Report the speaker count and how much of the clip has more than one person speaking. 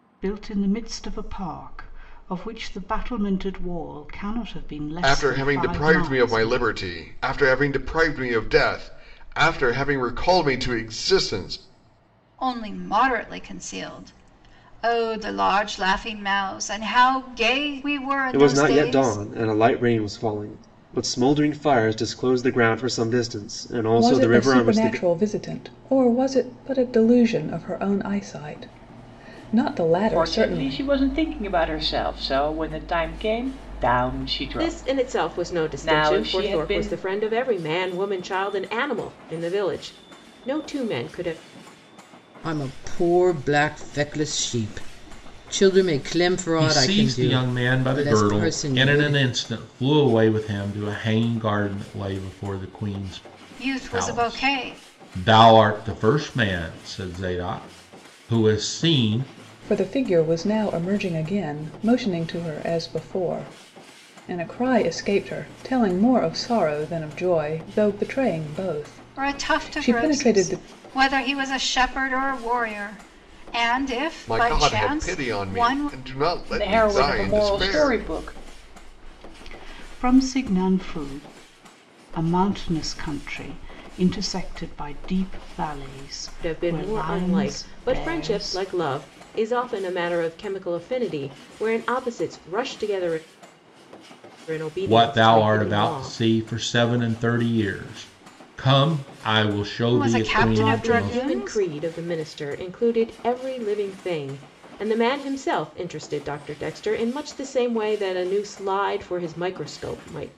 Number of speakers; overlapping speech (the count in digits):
9, about 19%